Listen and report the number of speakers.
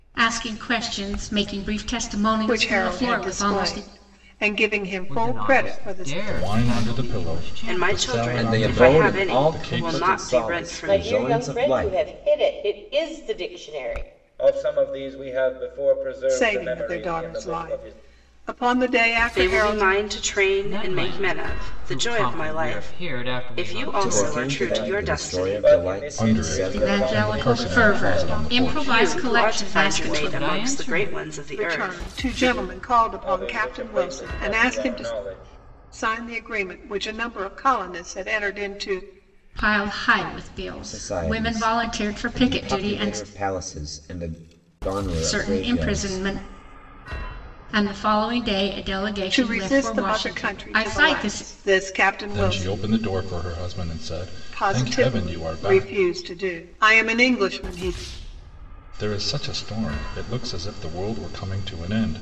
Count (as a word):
eight